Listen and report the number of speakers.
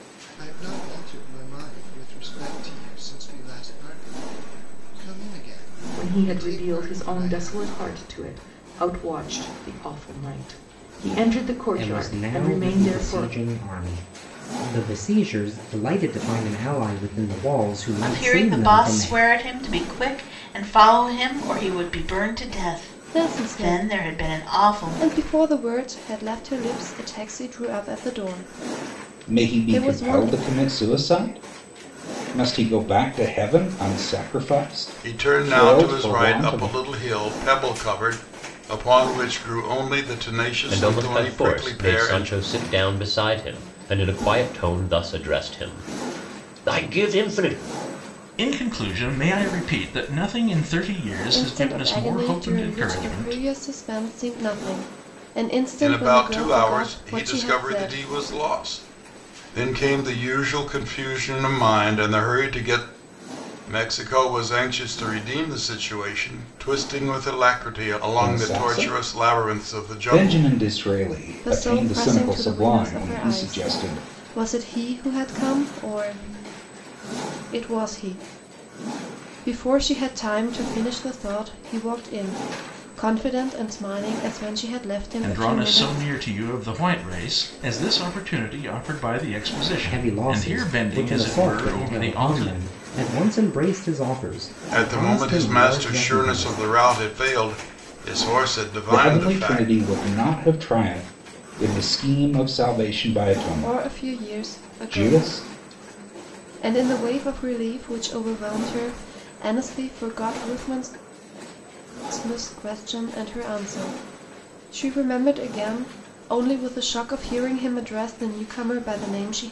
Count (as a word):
nine